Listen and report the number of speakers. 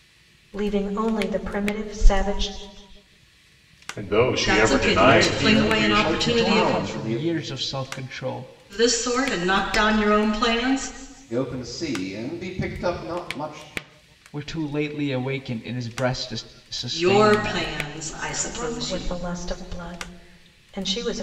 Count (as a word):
five